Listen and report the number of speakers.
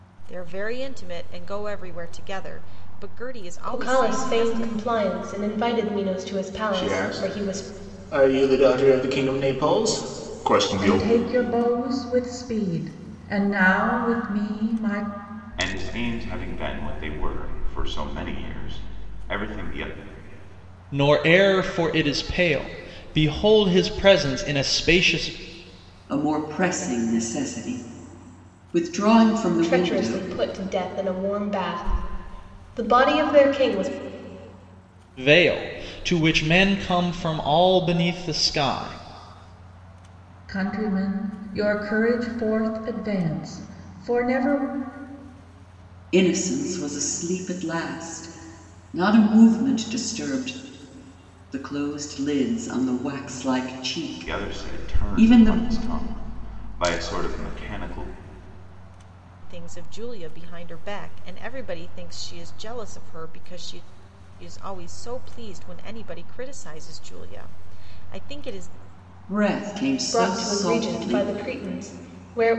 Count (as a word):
seven